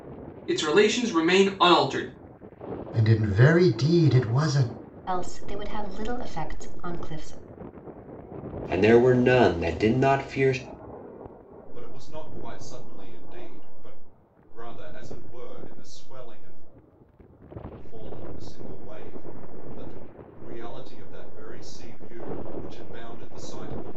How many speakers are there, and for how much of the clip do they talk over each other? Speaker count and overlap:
five, no overlap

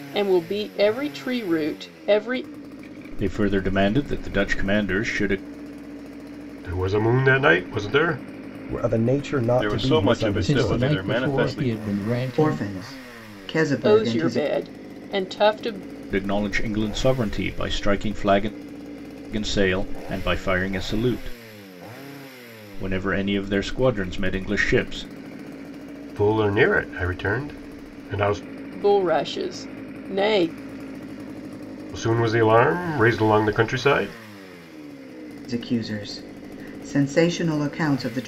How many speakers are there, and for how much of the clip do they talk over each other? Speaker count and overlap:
seven, about 8%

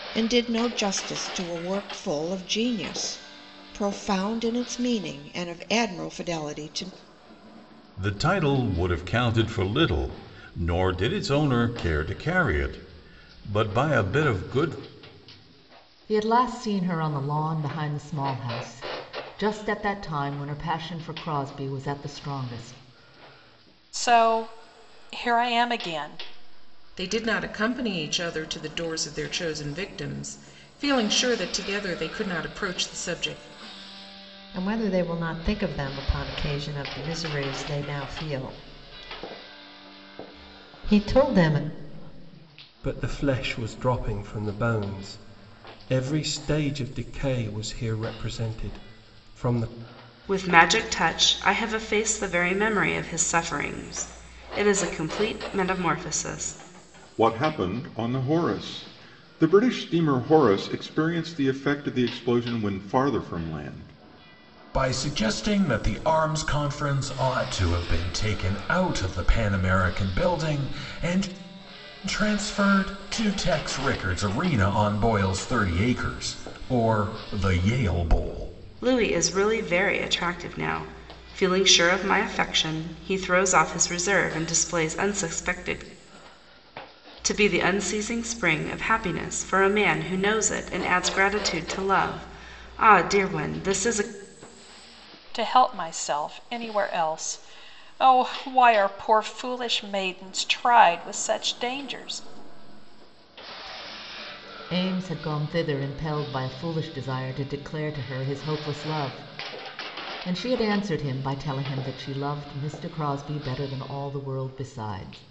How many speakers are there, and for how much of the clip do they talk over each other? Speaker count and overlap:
ten, no overlap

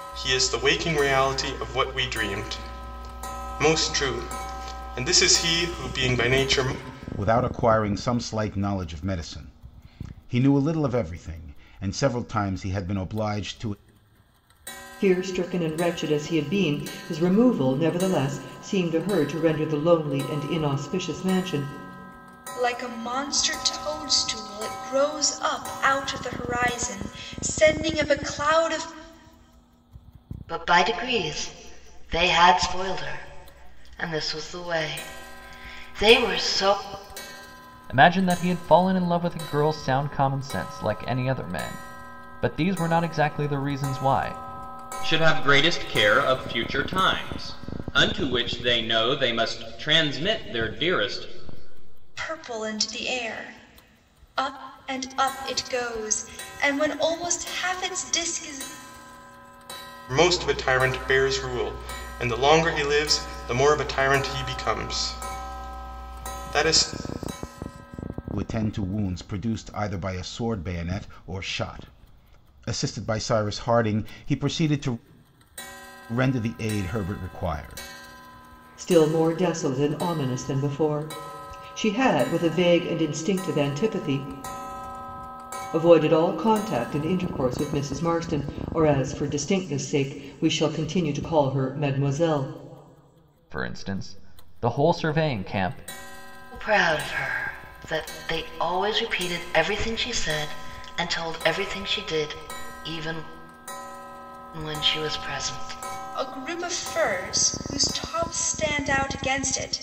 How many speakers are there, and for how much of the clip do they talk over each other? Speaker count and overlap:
seven, no overlap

